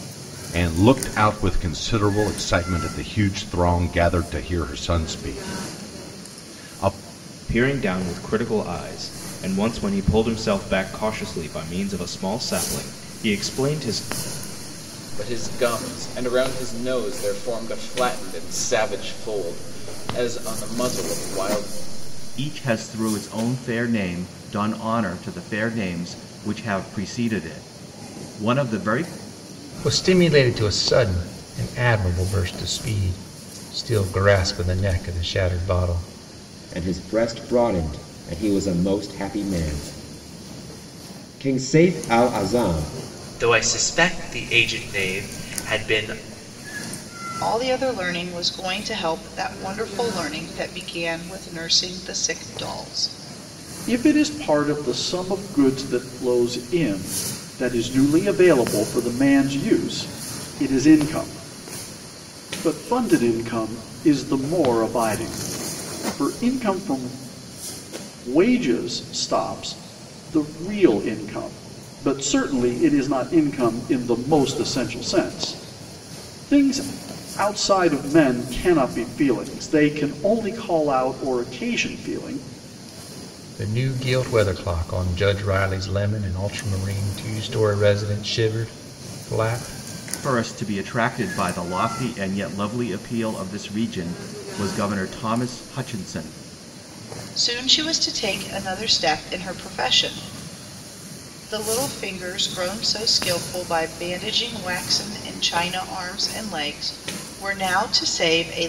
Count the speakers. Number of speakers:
nine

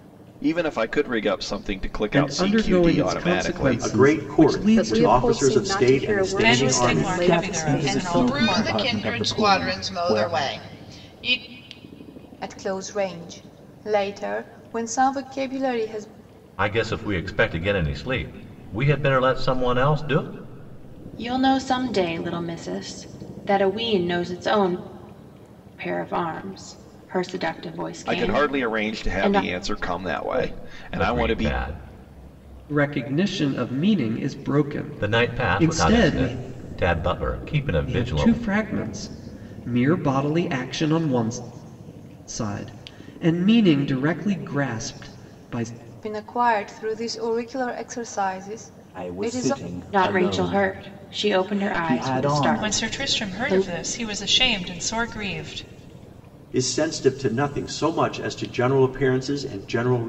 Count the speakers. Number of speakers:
ten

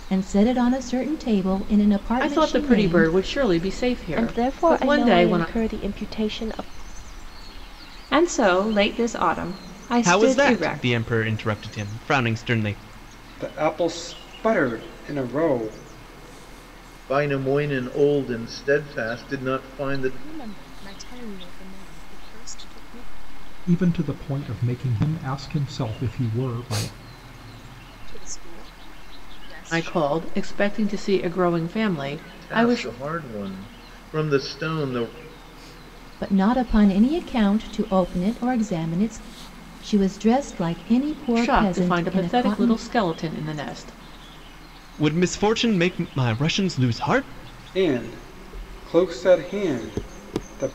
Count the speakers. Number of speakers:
nine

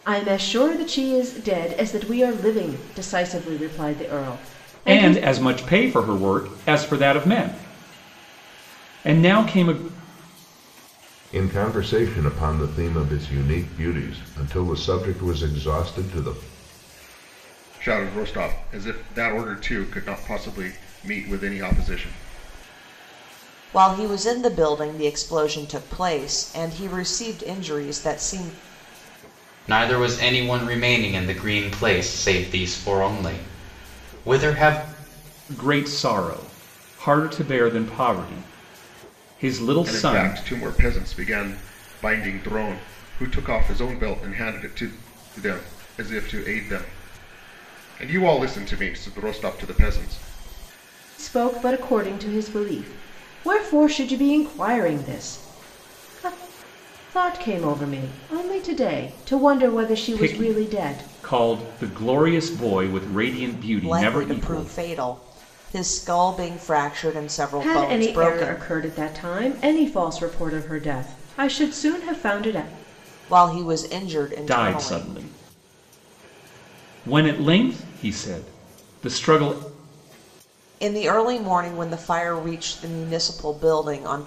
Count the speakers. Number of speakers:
six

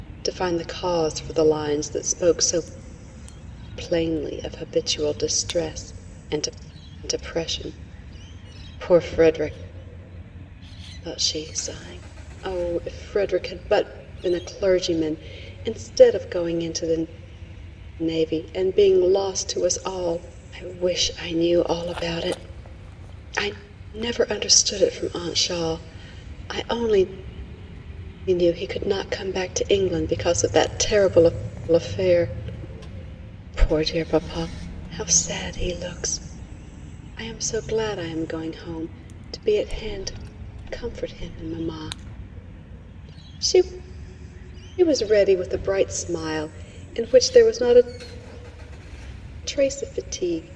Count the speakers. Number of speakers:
one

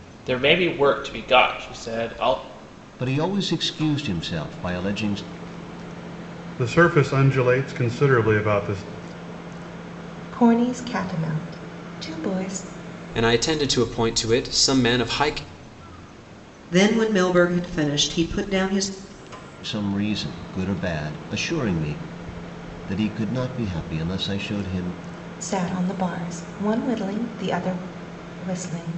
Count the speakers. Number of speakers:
six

